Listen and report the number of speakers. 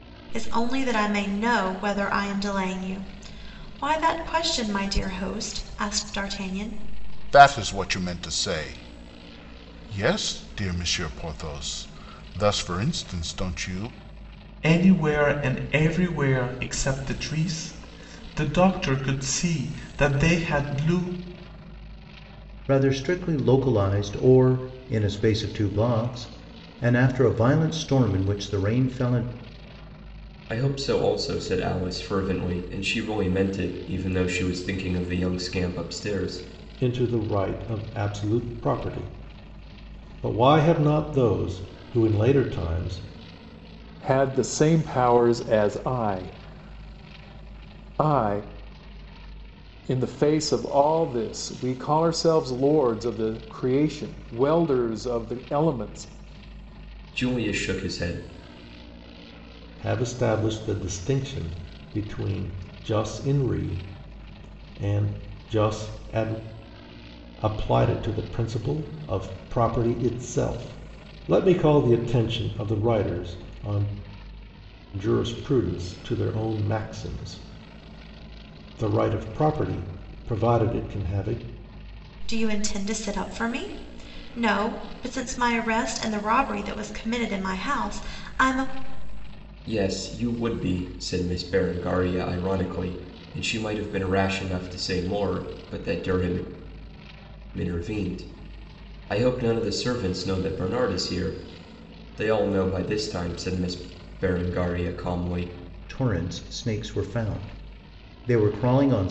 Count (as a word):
seven